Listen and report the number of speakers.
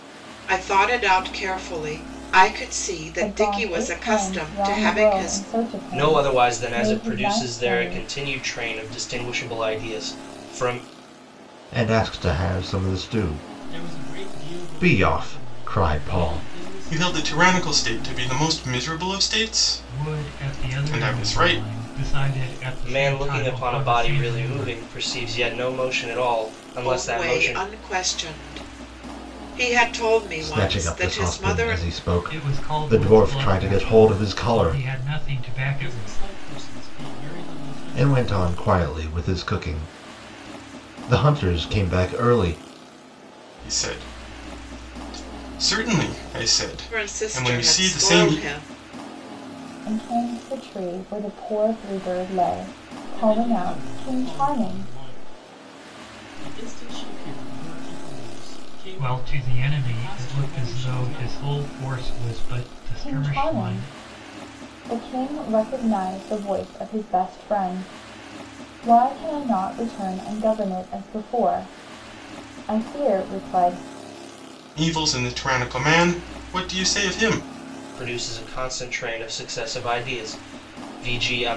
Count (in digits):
7